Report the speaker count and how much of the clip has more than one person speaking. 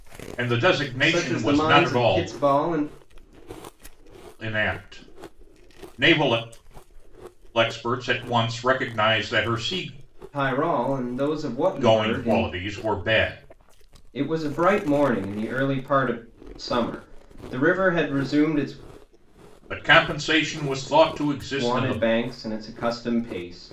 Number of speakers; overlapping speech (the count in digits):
2, about 11%